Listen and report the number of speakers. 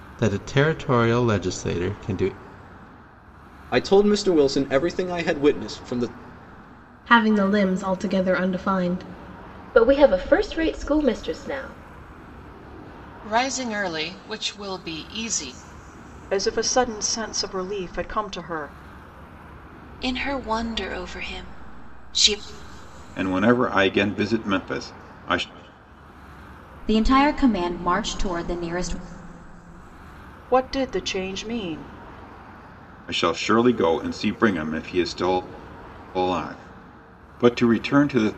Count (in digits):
9